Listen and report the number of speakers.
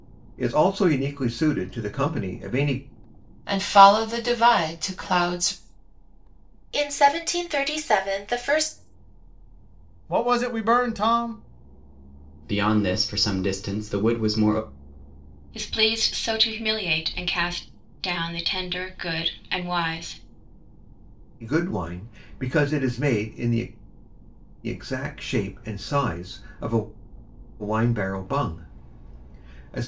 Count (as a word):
six